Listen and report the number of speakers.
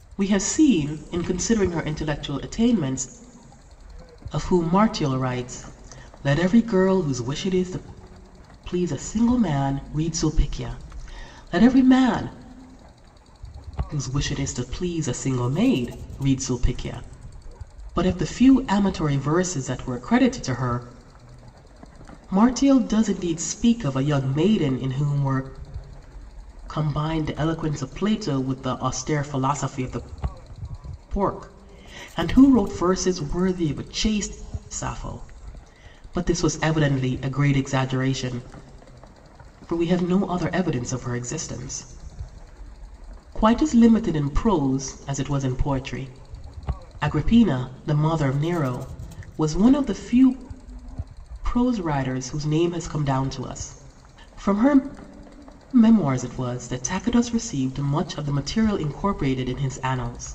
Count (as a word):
one